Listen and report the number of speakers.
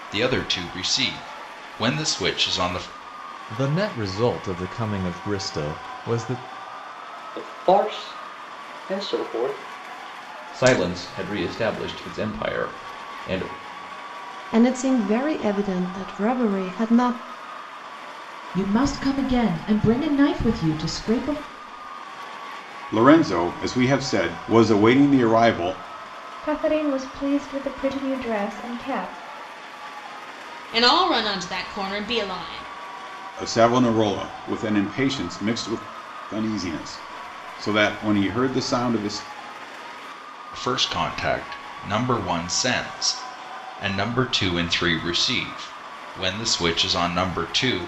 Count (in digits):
9